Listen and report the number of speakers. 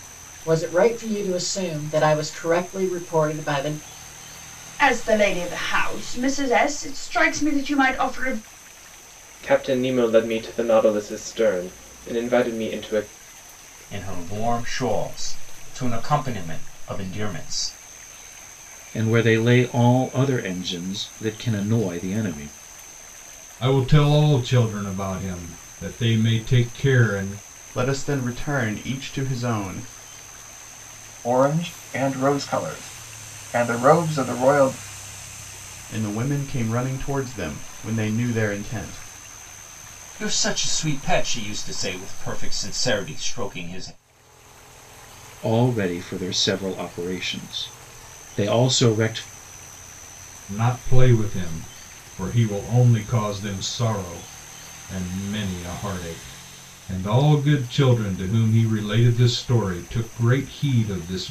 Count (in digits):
8